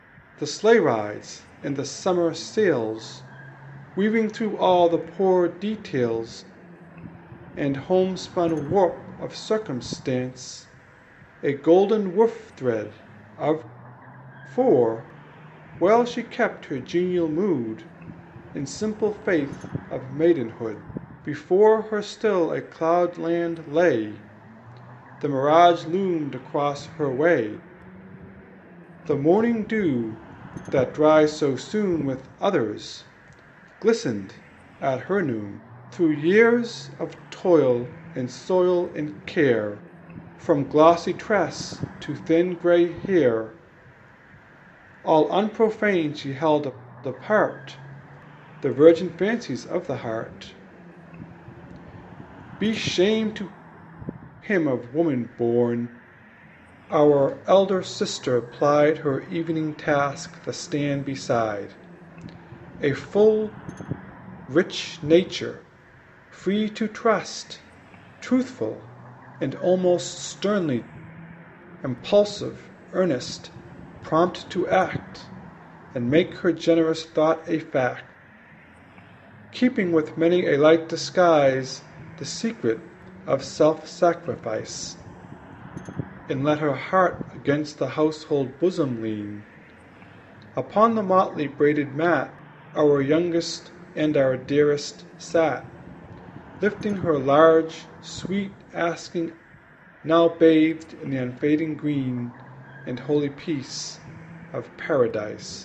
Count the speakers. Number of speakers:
1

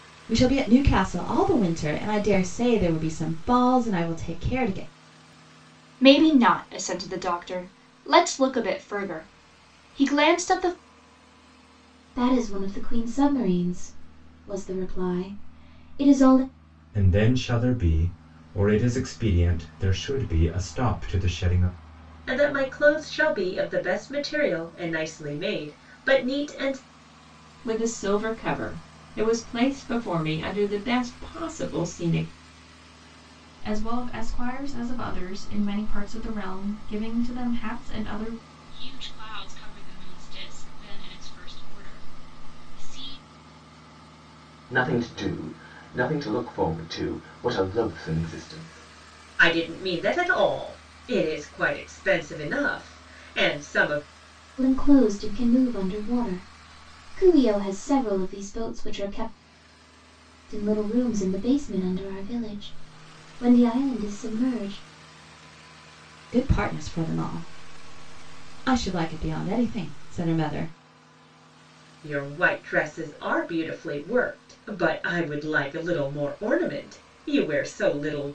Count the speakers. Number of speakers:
9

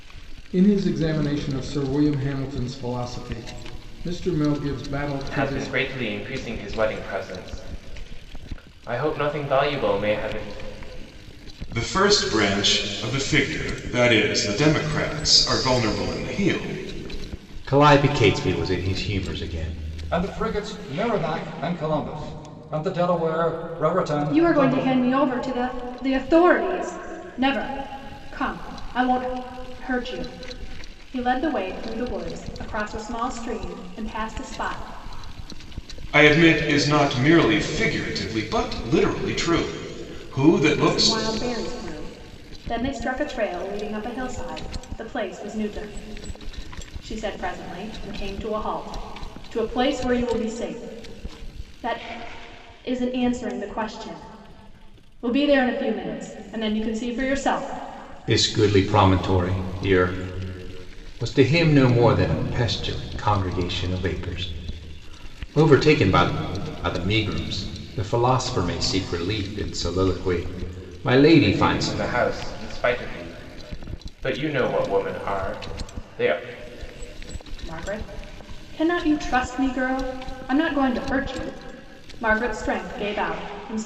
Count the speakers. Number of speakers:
6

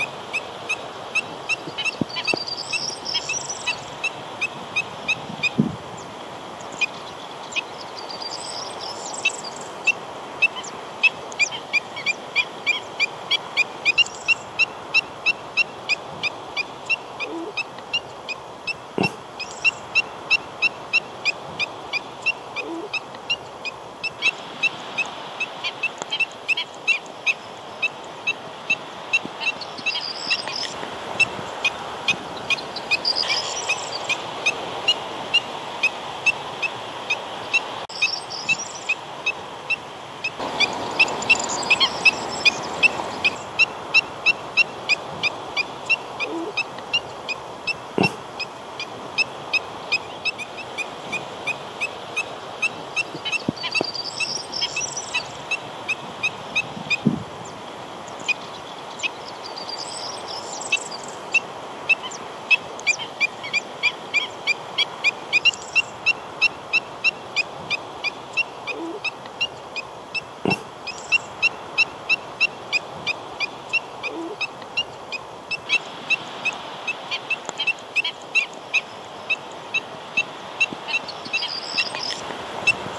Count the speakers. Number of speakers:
0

